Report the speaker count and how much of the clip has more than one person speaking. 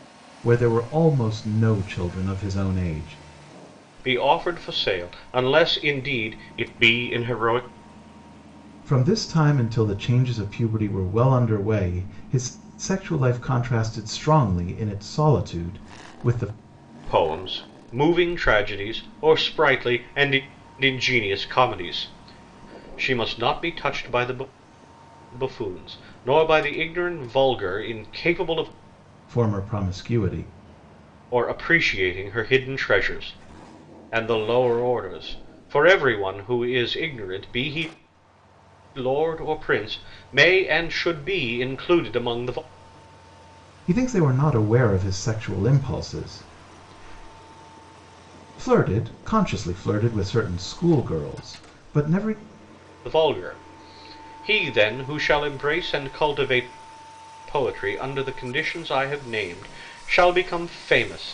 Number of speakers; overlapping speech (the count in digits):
2, no overlap